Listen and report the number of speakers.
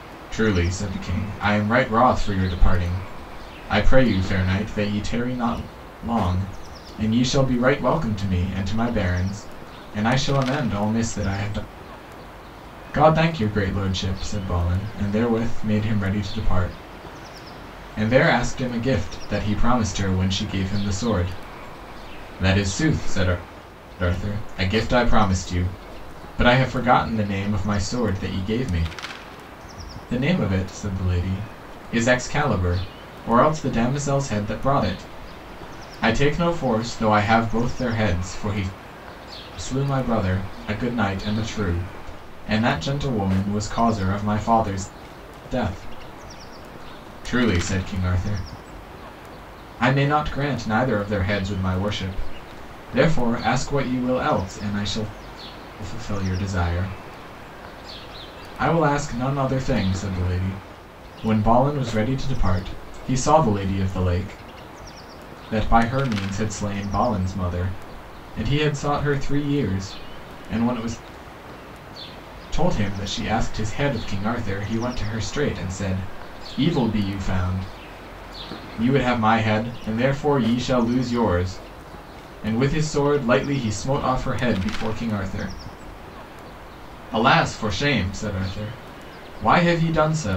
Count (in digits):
1